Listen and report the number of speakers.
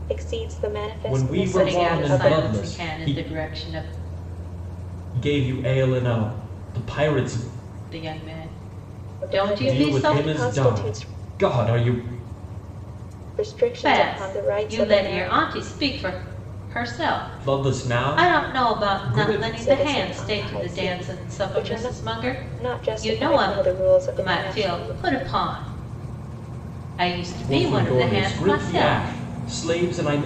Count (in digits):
3